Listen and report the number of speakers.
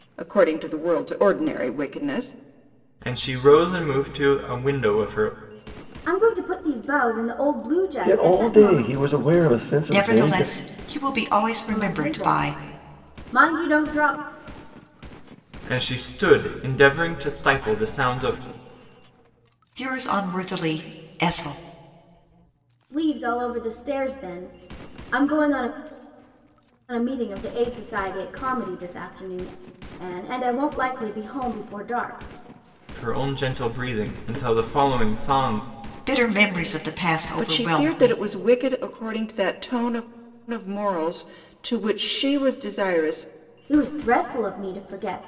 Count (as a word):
five